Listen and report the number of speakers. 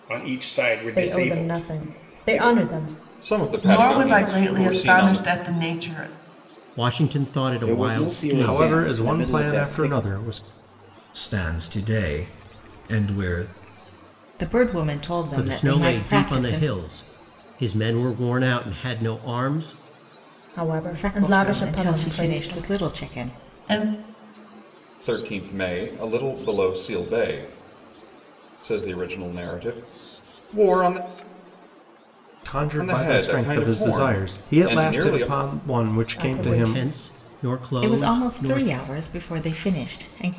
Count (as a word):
nine